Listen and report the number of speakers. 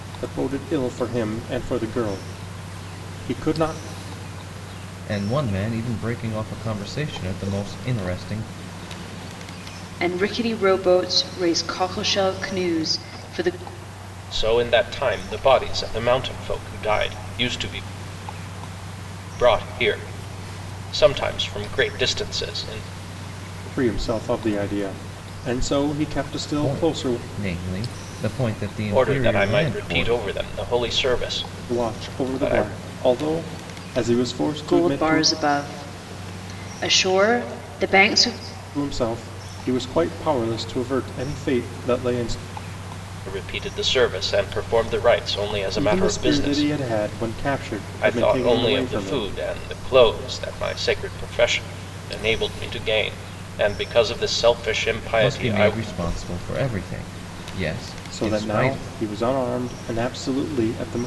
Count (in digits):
4